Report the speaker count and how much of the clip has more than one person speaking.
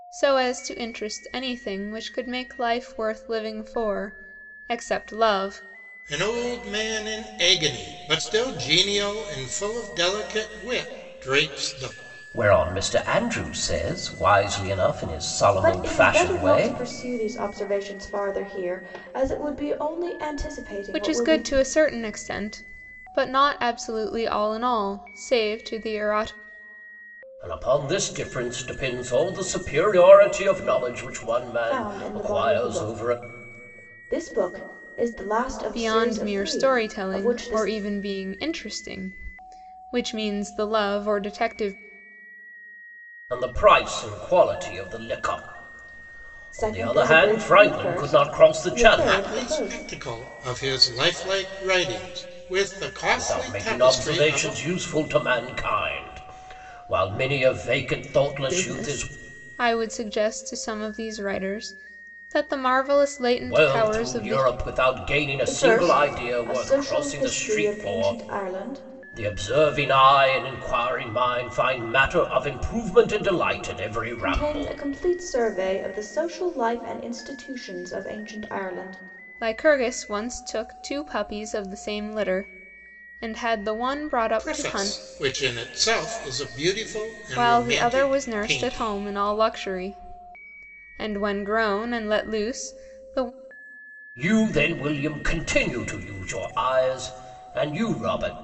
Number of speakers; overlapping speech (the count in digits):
4, about 18%